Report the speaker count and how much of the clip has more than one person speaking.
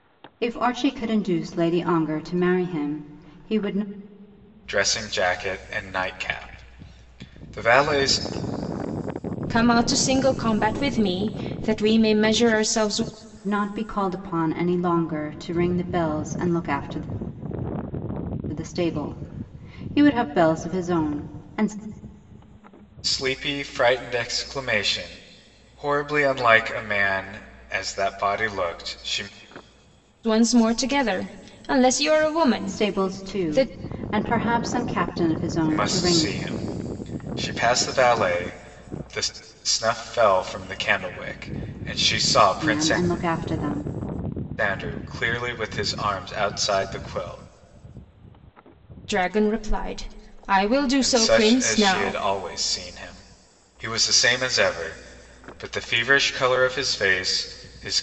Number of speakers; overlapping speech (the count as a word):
three, about 6%